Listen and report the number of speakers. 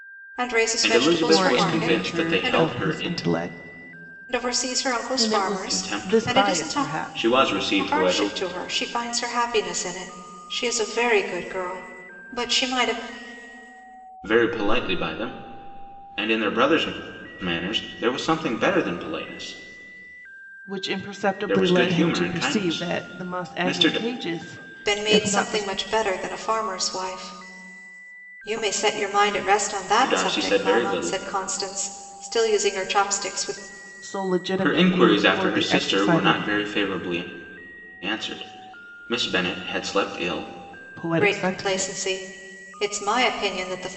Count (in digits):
3